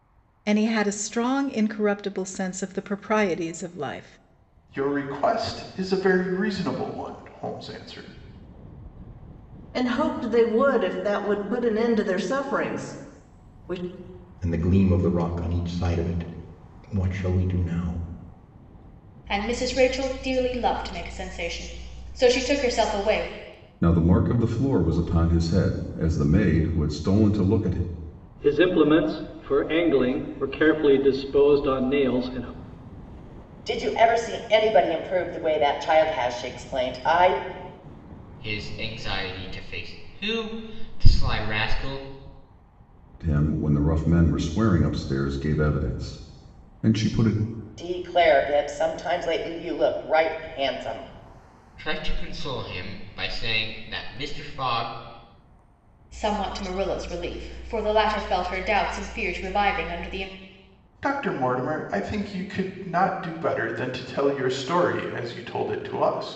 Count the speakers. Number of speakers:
nine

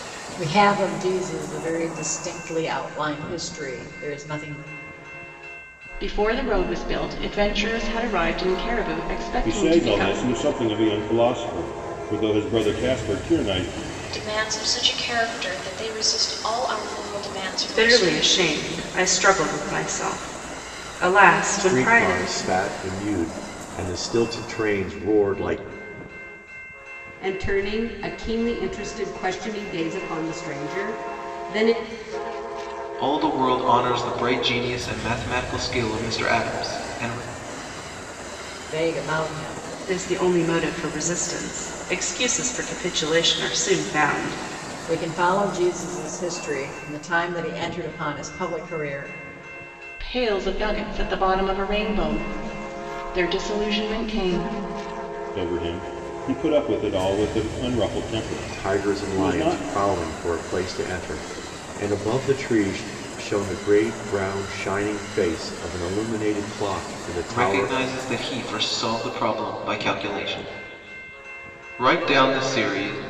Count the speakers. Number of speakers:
eight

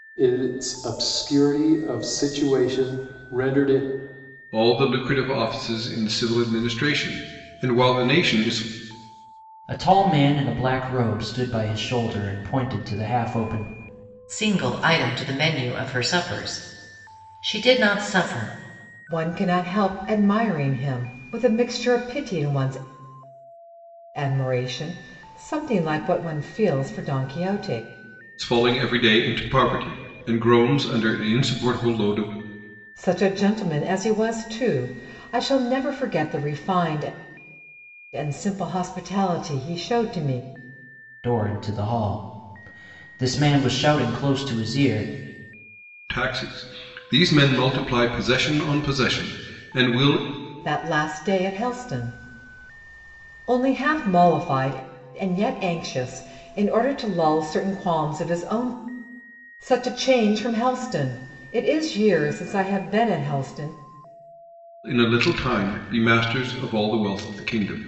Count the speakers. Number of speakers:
five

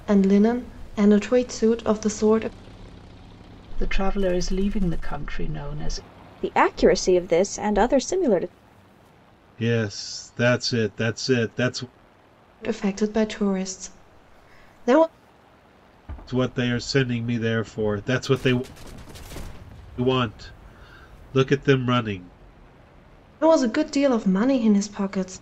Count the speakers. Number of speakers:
four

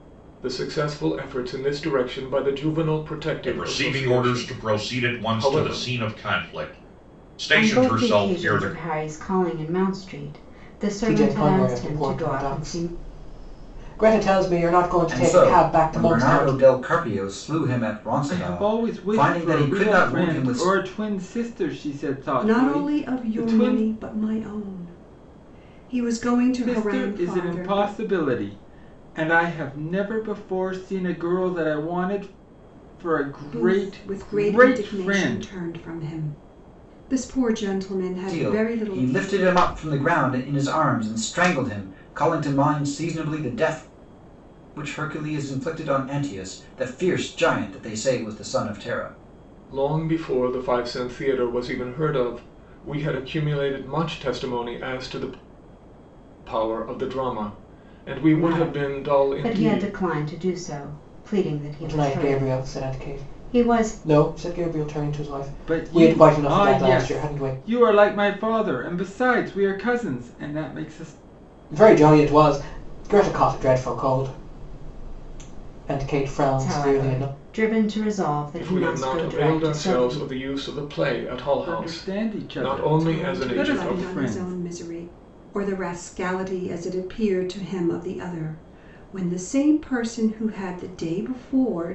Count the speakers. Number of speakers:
seven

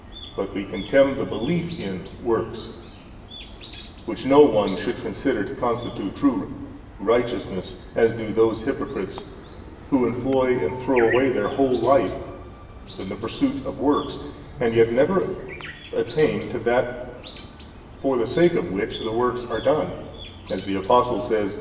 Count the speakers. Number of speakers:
one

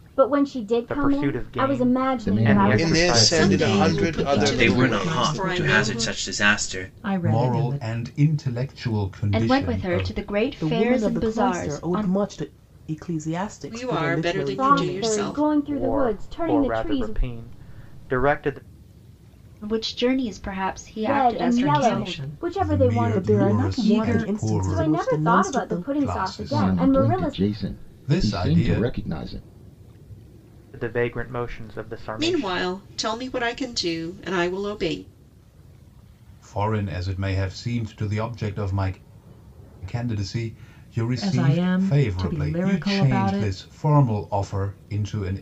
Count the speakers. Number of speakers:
ten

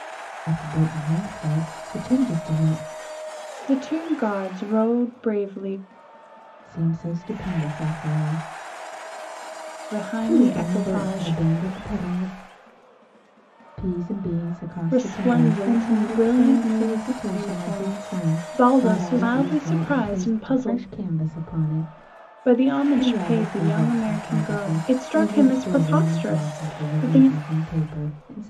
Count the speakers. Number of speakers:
two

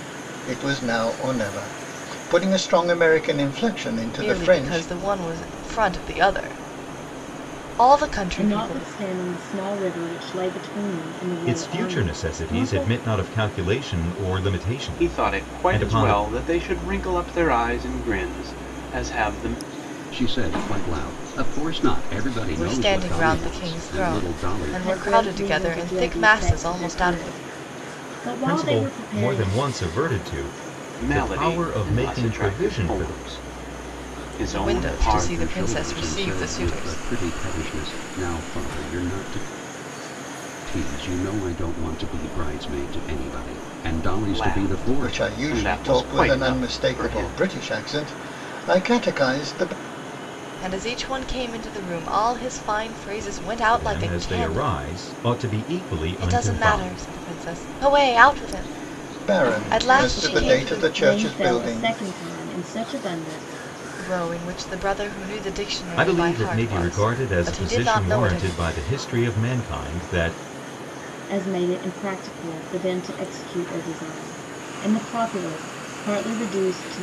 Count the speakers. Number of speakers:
six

